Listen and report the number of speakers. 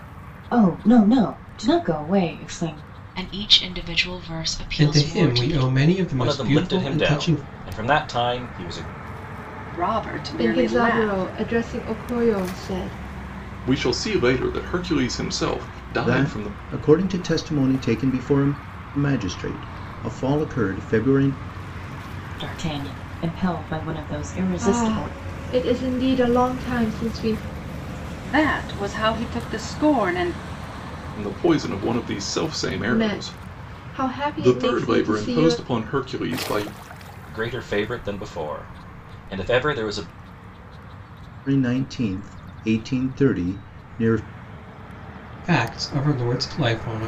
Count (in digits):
8